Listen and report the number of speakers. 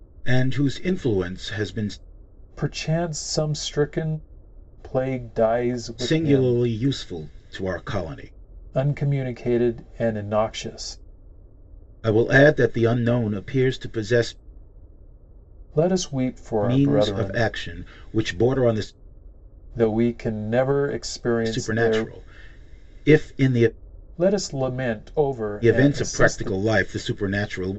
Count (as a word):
two